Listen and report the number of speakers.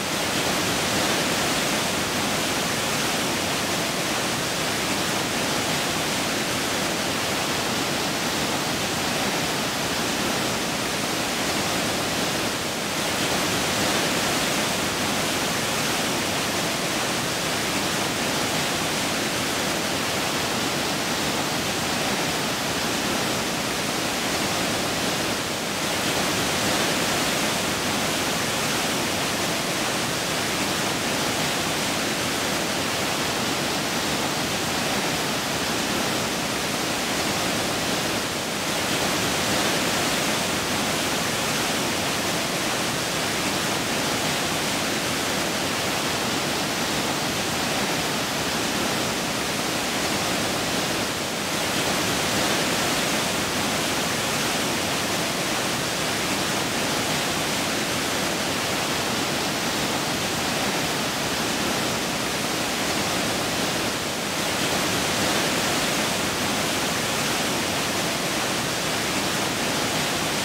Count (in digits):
0